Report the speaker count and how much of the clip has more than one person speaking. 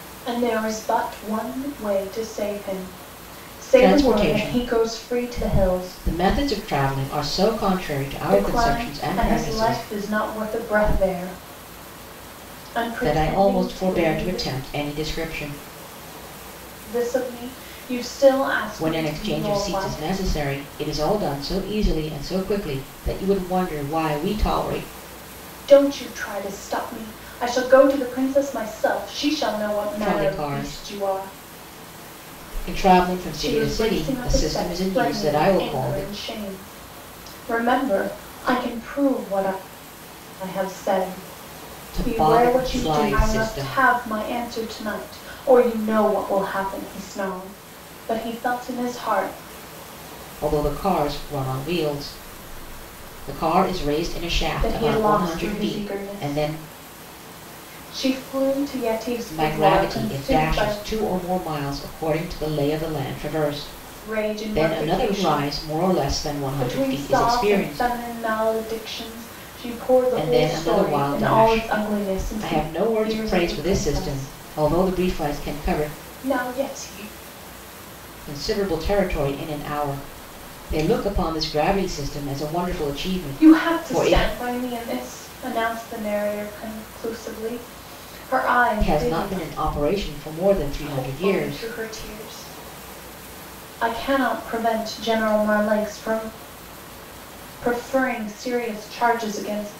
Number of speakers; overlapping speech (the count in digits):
2, about 27%